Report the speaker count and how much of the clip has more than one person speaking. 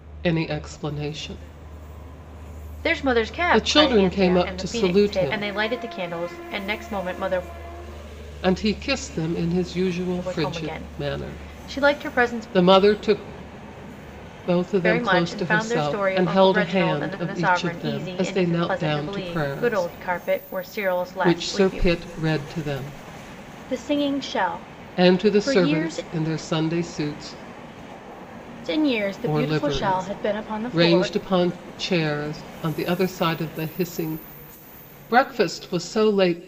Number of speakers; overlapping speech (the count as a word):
two, about 36%